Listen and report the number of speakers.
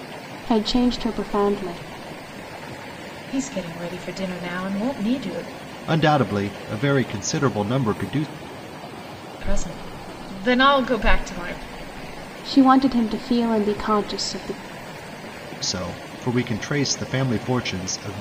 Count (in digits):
3